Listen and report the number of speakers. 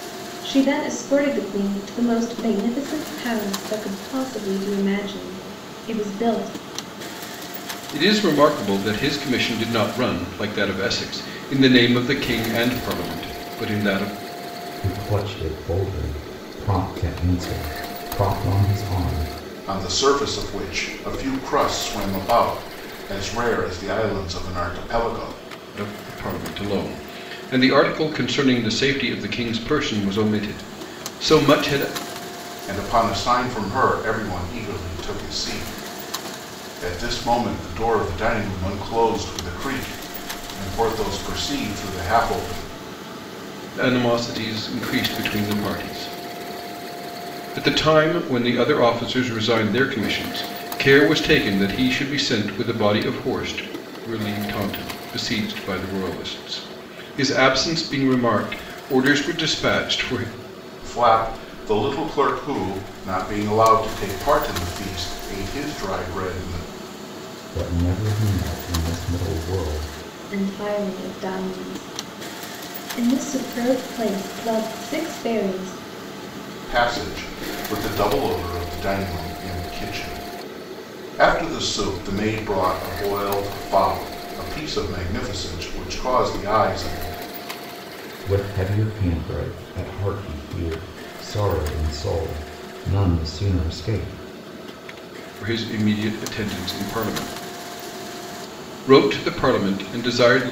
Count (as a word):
four